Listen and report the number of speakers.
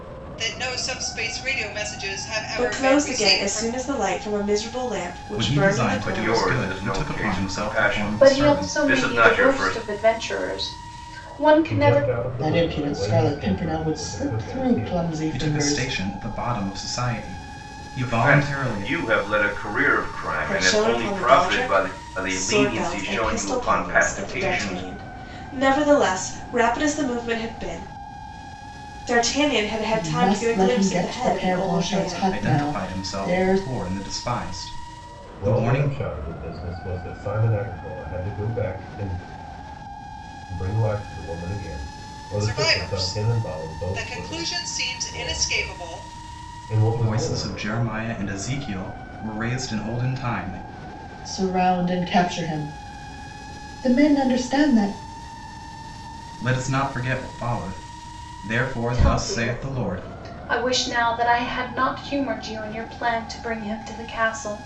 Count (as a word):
seven